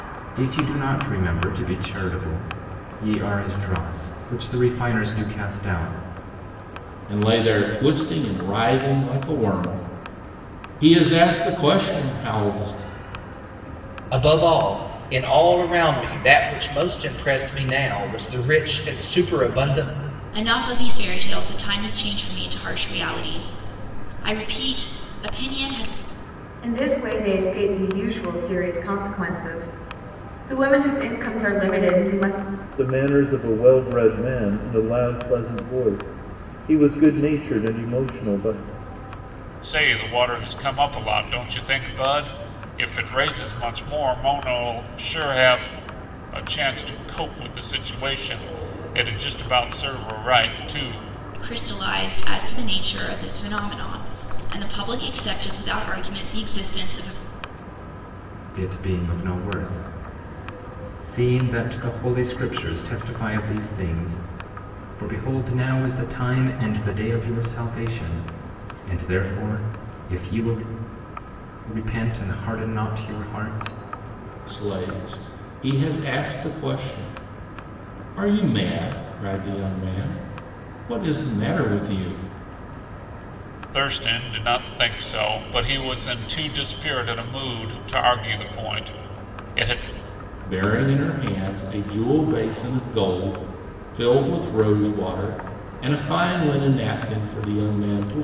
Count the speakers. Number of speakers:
seven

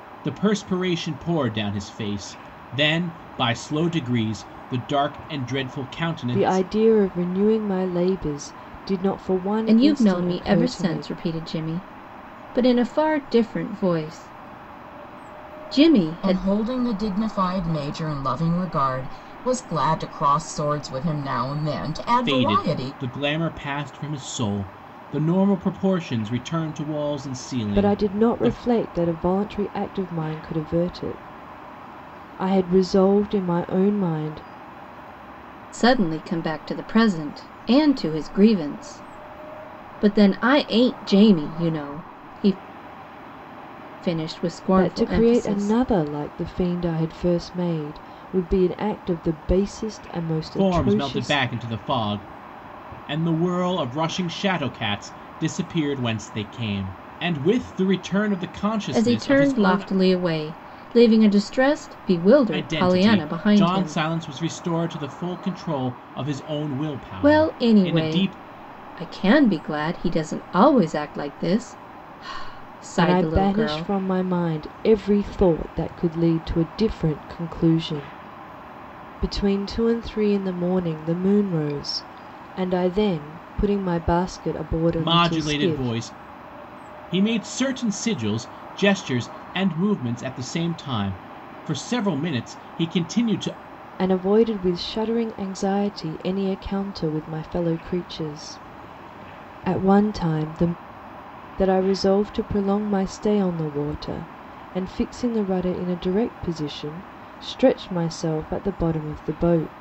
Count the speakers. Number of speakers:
four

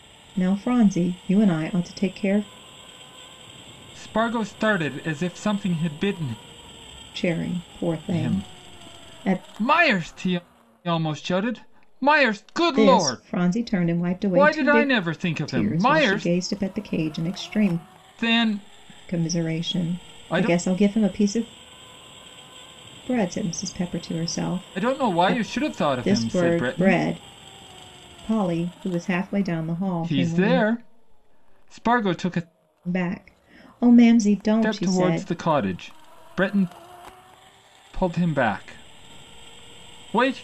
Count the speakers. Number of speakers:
two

